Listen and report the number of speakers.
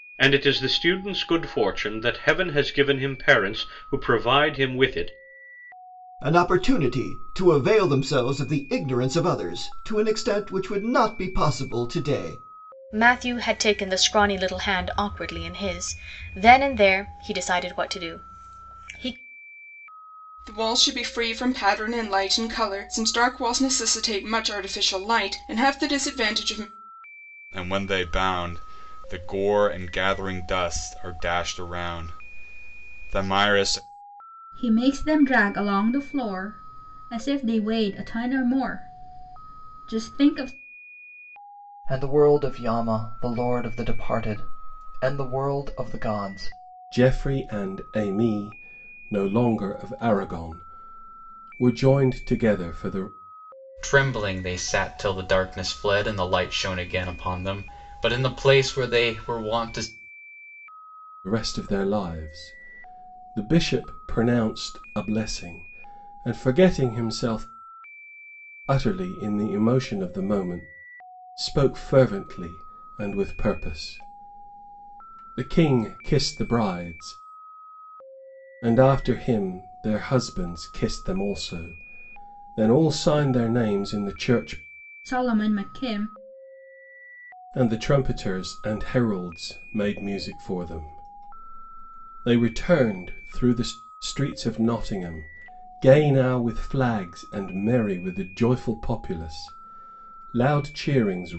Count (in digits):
9